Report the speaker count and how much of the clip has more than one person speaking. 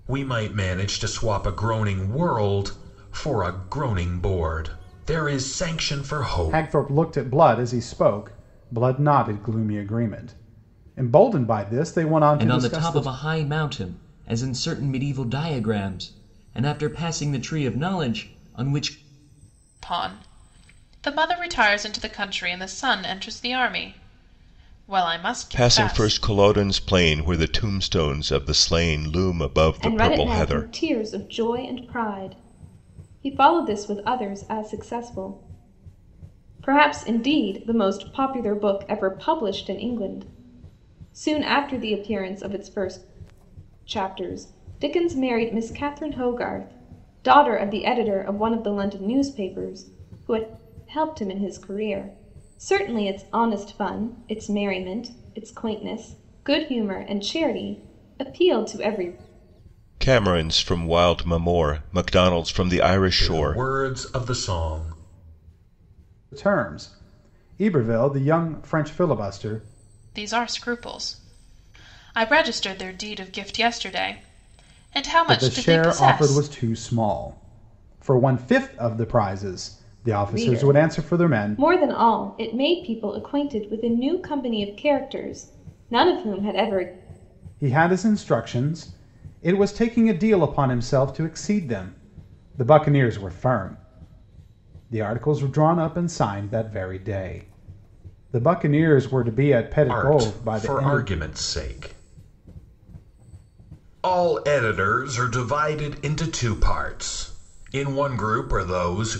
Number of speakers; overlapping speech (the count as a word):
six, about 6%